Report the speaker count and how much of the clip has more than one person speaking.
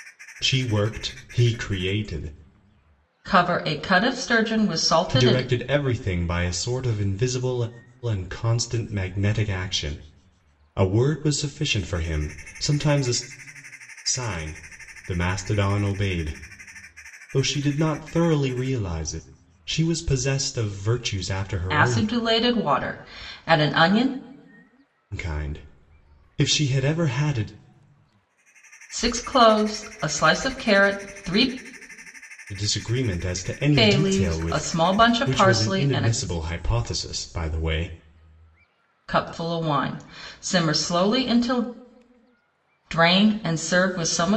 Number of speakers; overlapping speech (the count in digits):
2, about 6%